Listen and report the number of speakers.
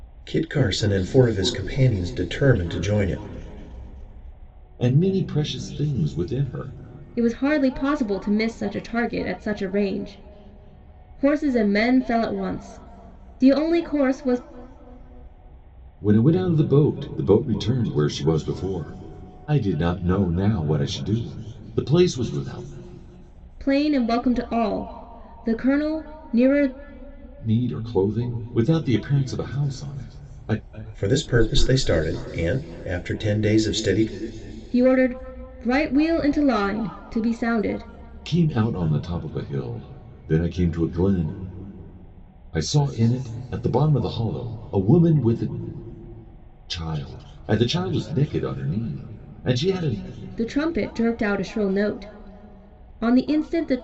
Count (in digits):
3